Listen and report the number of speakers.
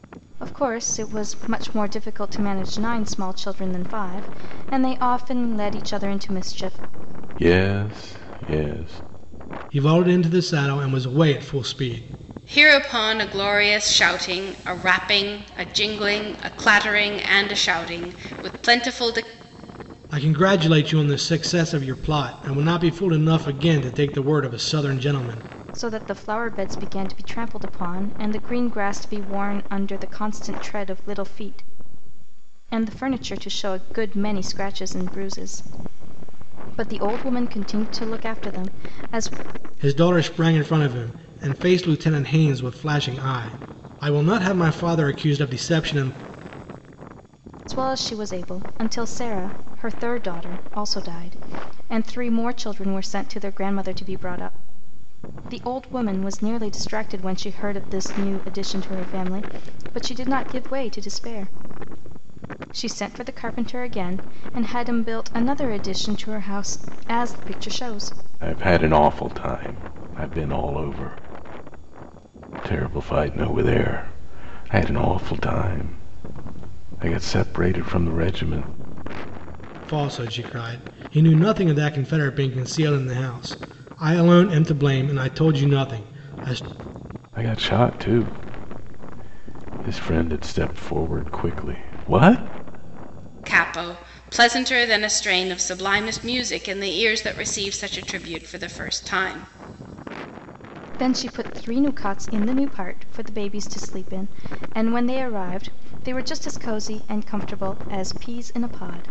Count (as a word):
four